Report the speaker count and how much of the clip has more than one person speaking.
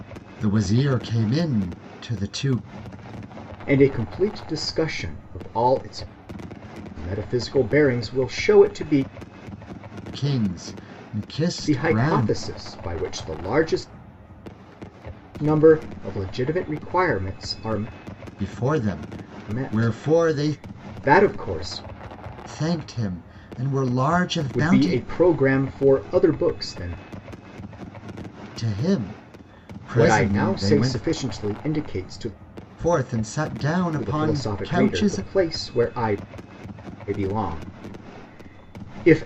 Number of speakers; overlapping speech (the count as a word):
two, about 12%